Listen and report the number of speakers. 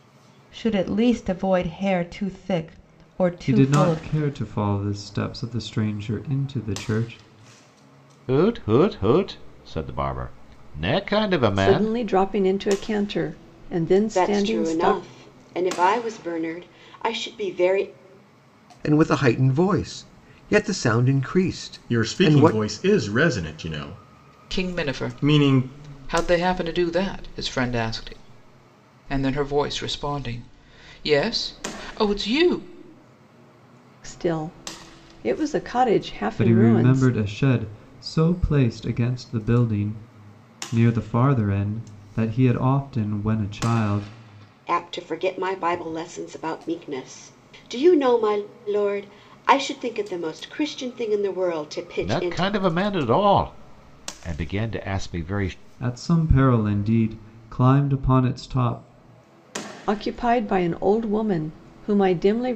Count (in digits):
8